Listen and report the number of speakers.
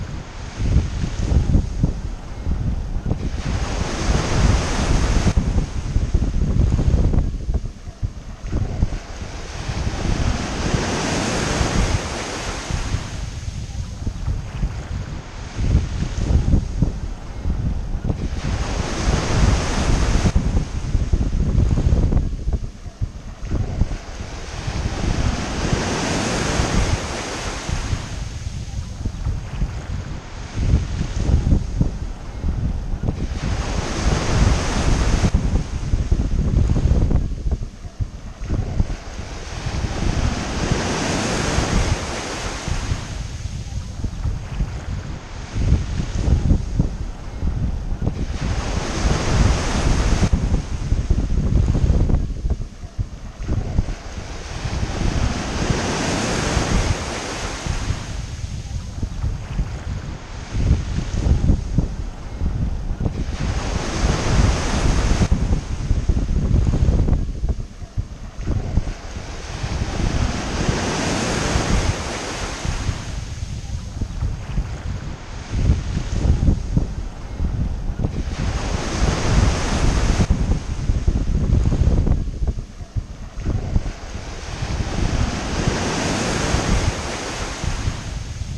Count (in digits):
0